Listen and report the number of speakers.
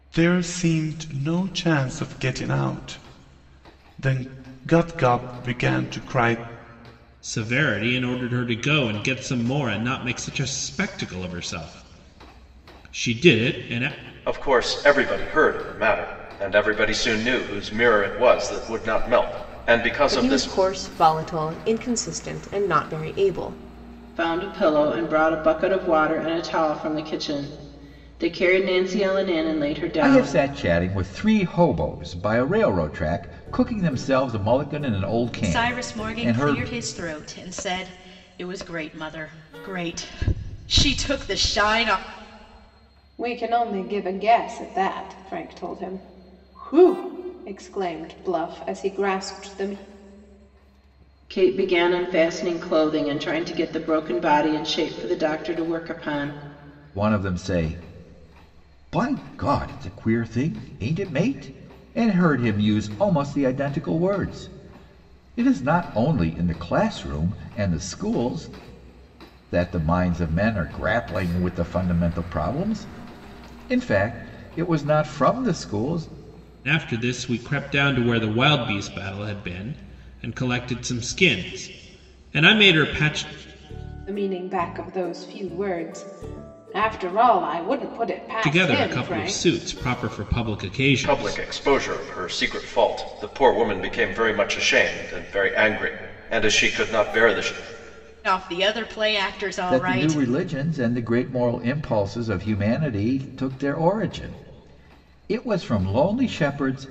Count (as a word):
eight